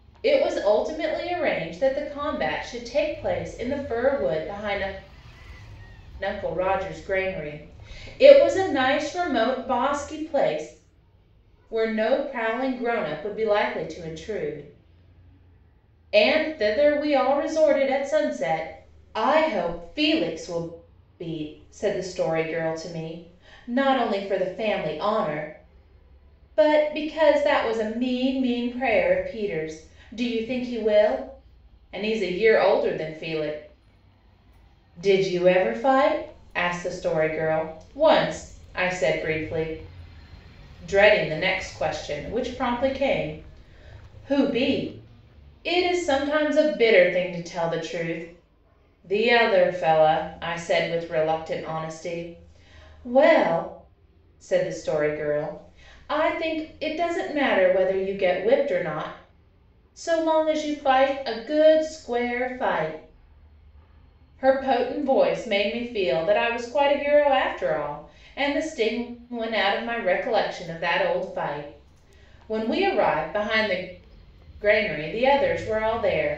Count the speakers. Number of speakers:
one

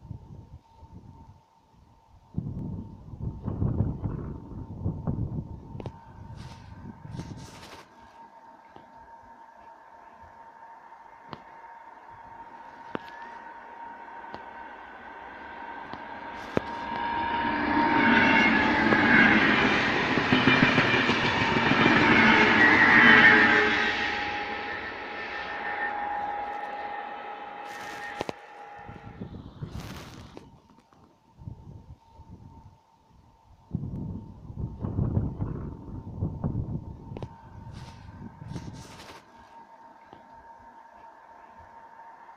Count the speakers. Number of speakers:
zero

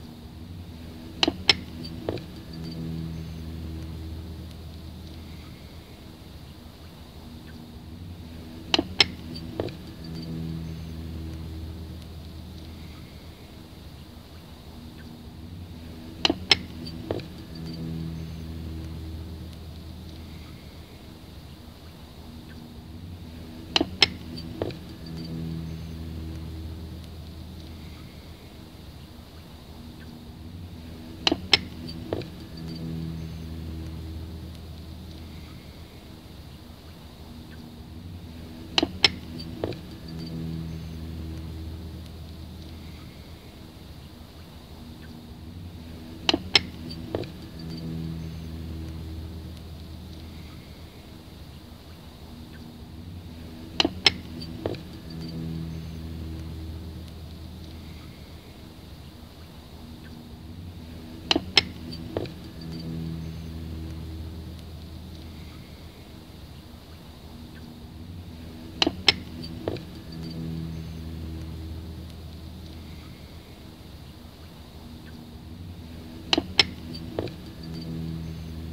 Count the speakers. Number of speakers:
zero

